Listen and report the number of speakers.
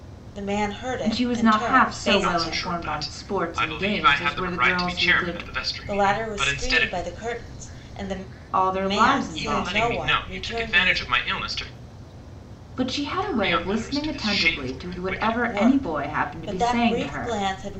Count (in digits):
3